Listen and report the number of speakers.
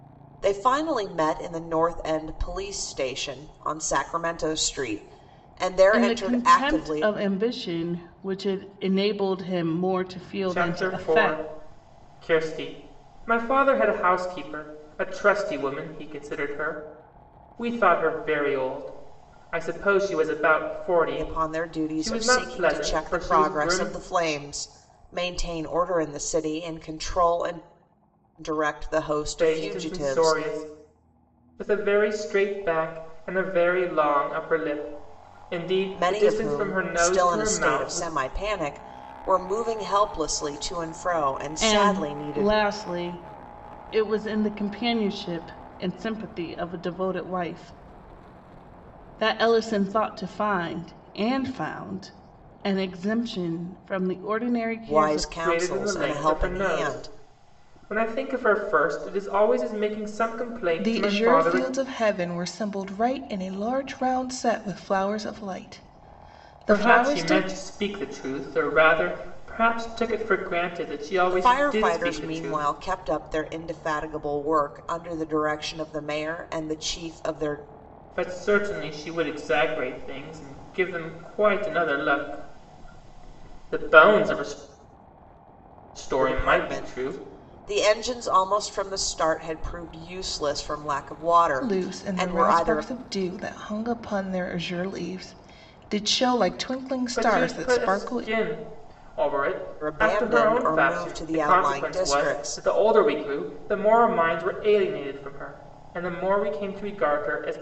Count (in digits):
3